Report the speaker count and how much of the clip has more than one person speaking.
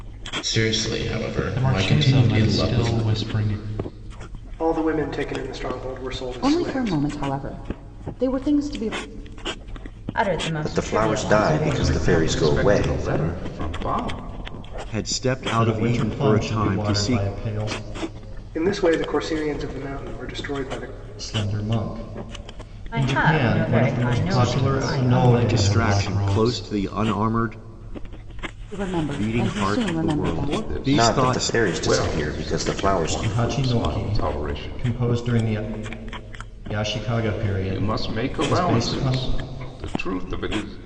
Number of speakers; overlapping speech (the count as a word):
ten, about 44%